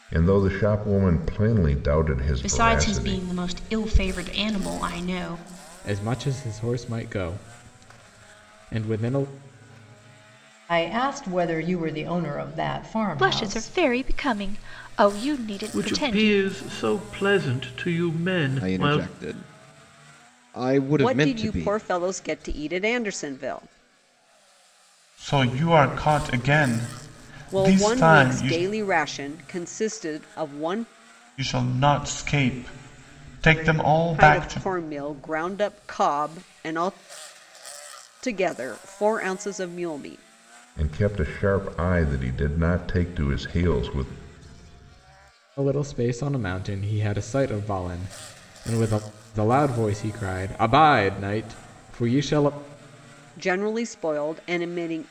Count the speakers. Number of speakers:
9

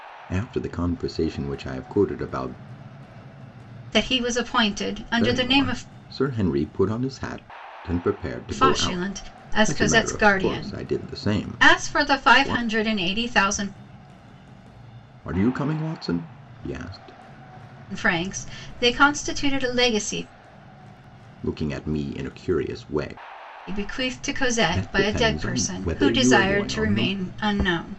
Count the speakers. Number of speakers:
2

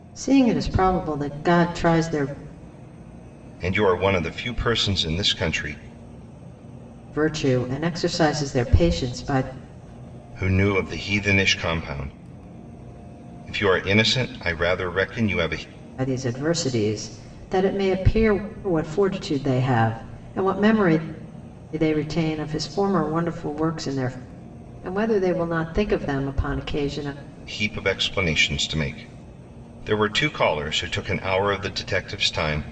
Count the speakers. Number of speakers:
2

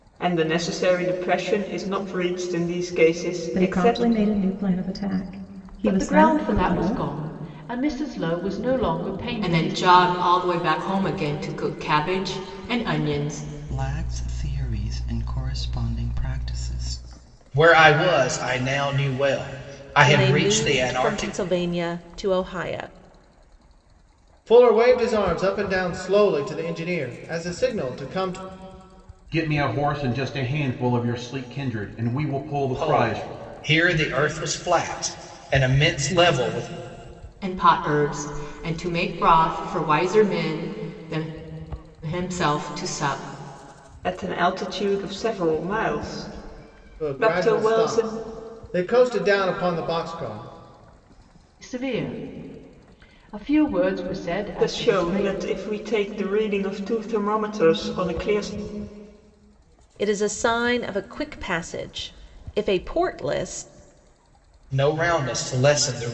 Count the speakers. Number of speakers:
9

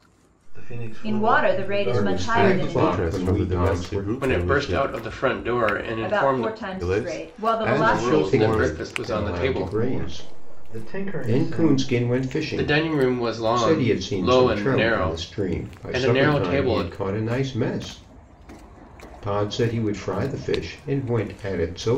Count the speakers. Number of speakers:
5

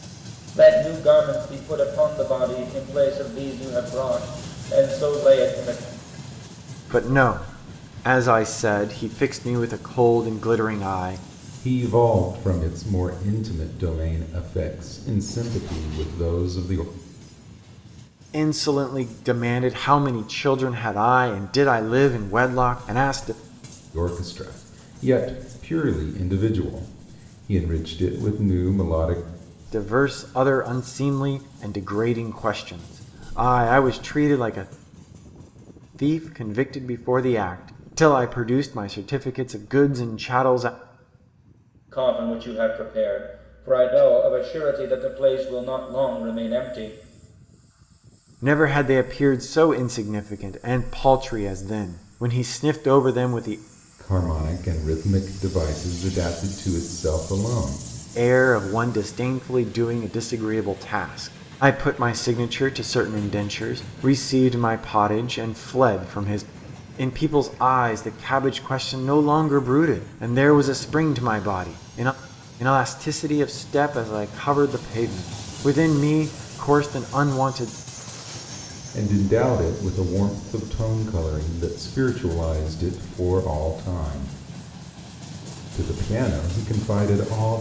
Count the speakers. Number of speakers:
3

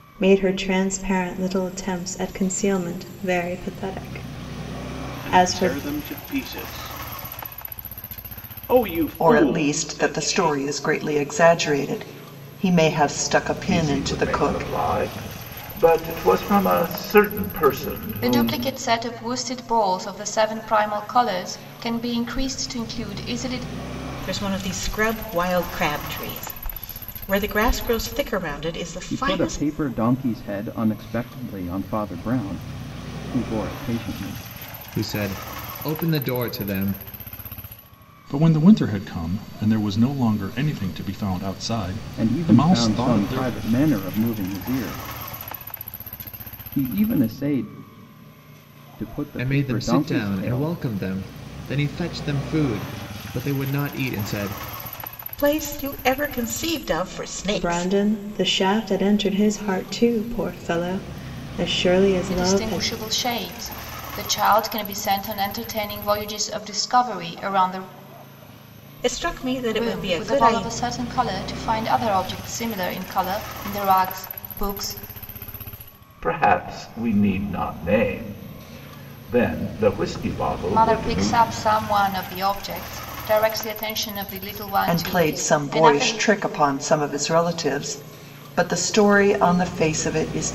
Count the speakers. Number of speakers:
9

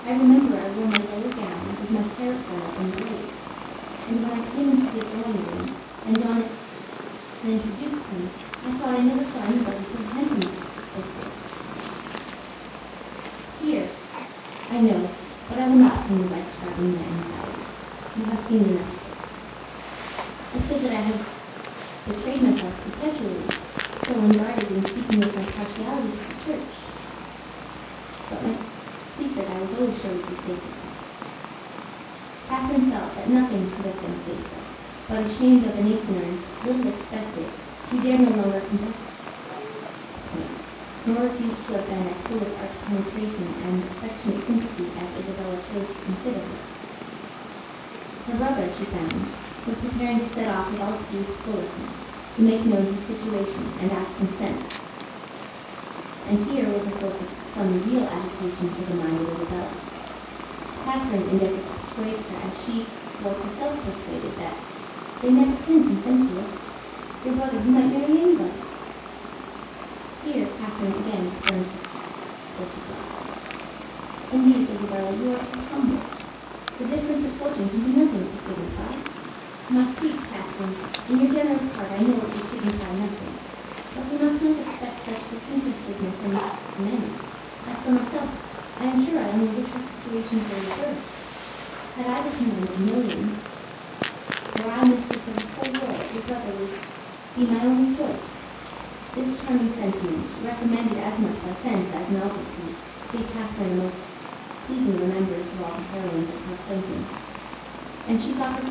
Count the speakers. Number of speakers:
1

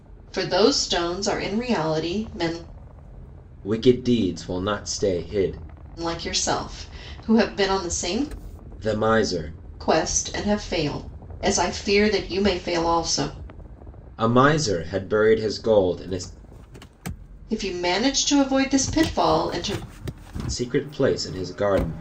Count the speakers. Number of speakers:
2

